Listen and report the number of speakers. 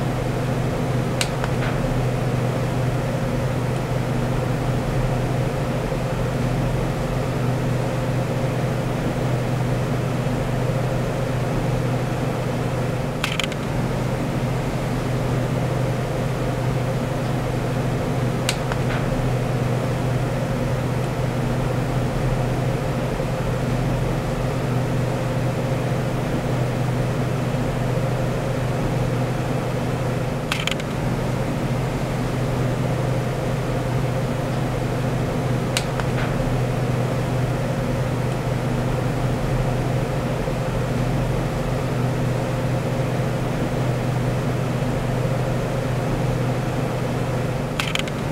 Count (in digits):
0